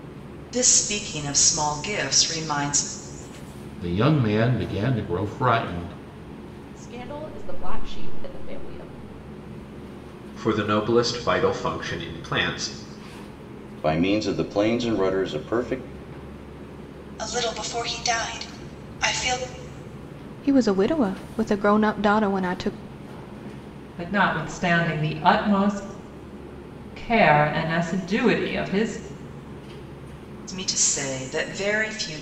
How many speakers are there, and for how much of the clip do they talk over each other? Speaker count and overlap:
8, no overlap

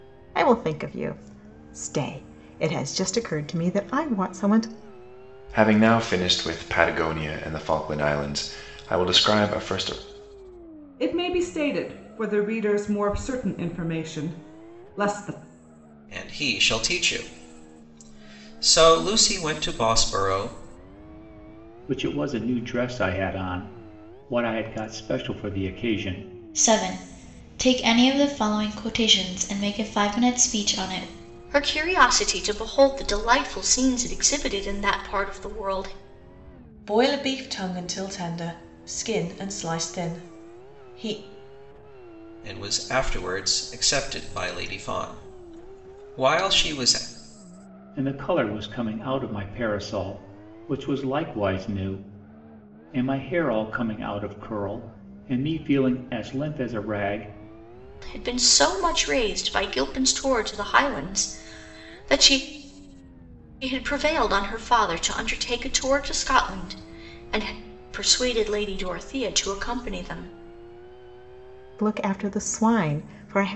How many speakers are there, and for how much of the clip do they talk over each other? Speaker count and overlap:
8, no overlap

